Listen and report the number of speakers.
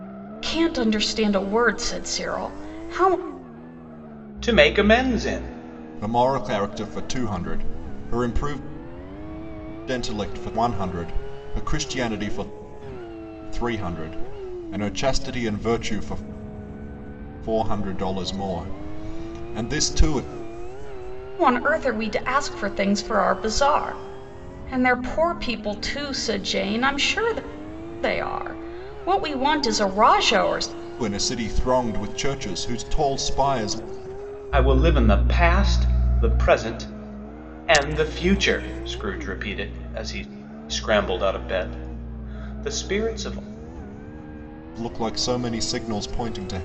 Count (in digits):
3